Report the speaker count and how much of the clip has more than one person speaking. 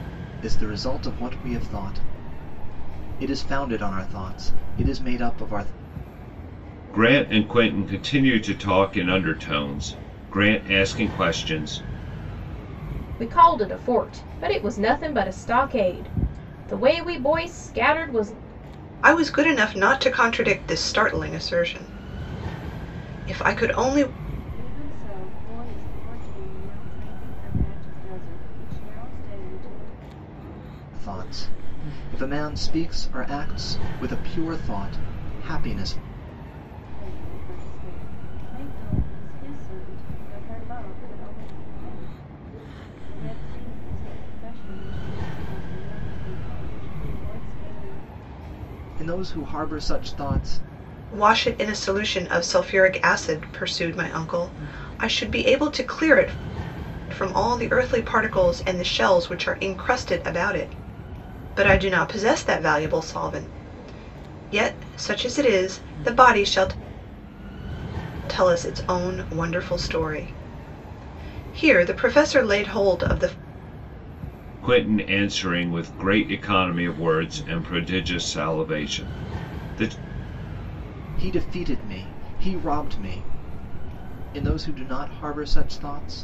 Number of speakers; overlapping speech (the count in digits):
5, no overlap